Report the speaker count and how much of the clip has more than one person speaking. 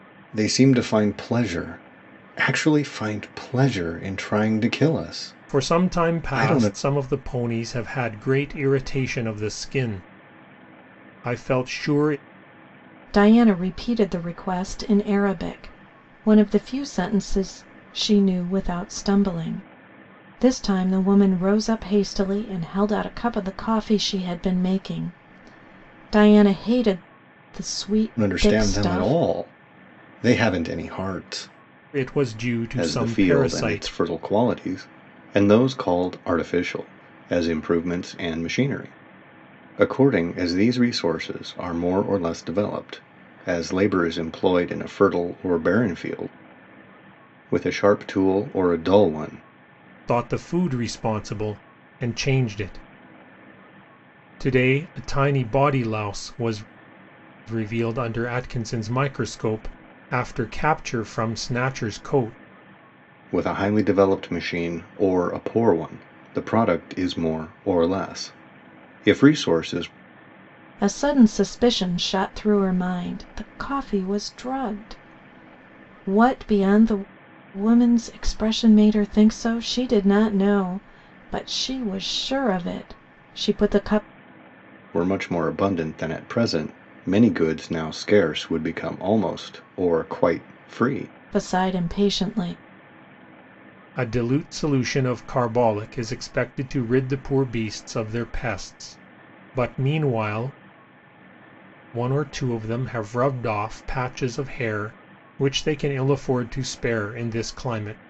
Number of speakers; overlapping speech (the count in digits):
3, about 3%